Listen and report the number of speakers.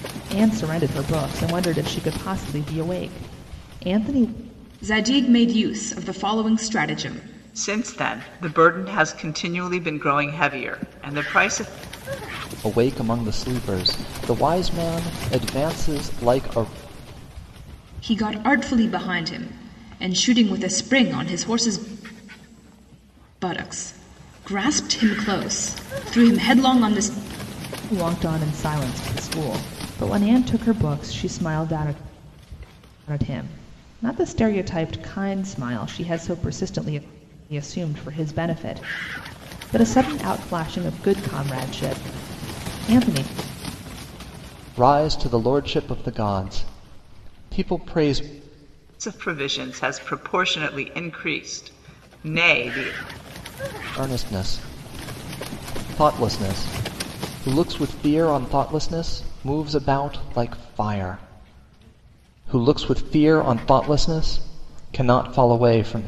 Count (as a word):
four